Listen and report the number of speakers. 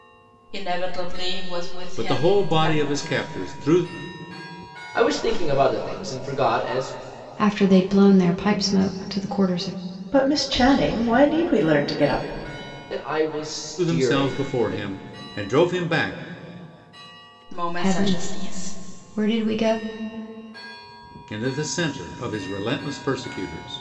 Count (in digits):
5